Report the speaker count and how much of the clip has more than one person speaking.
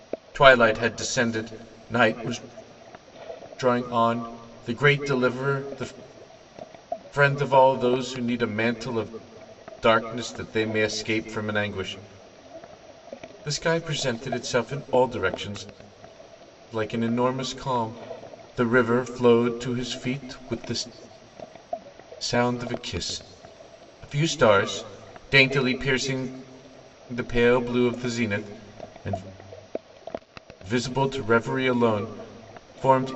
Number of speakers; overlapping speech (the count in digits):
1, no overlap